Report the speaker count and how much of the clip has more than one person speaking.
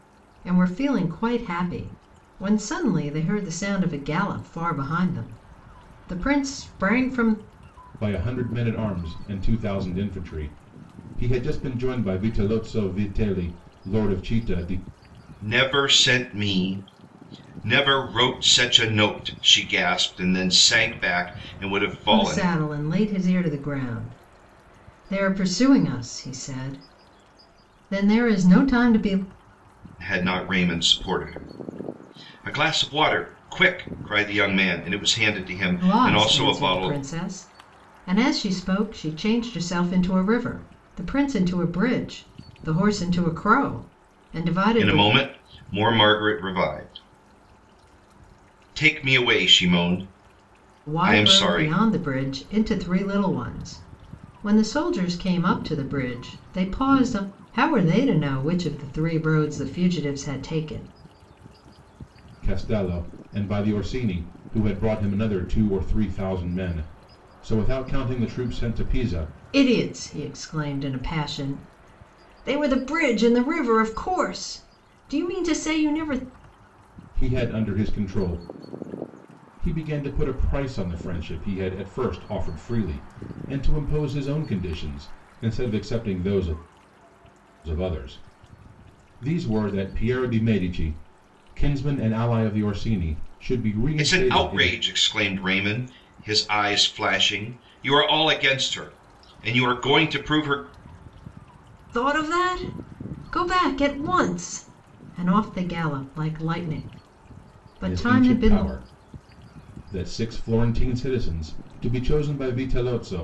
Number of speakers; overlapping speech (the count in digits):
3, about 4%